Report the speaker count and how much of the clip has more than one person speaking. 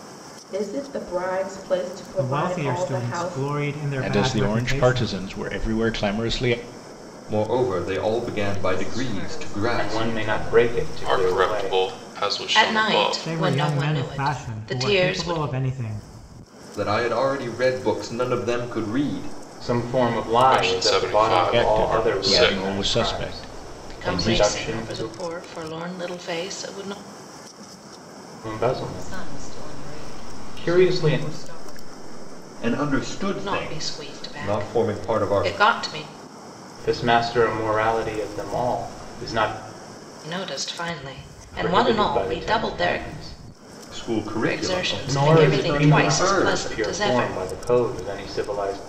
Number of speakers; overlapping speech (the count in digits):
8, about 46%